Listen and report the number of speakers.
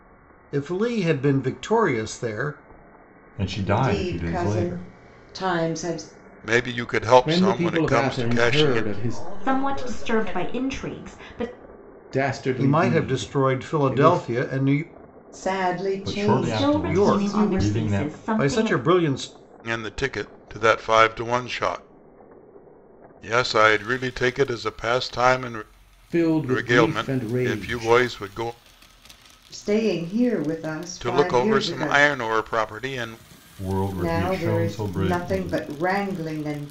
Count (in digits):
7